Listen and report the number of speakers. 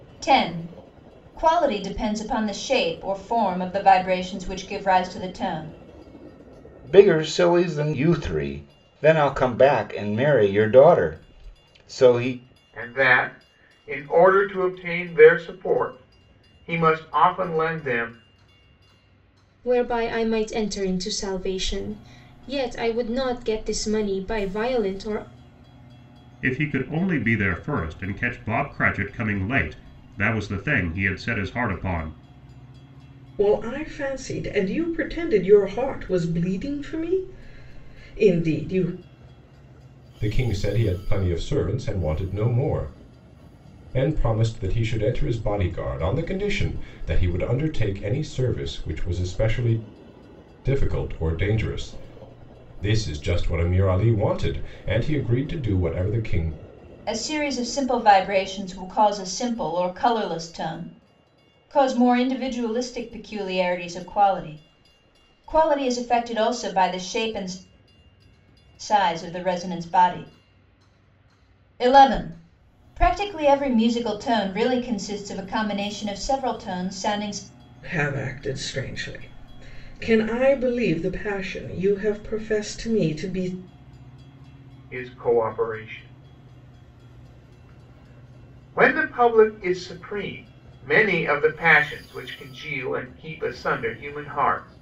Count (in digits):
7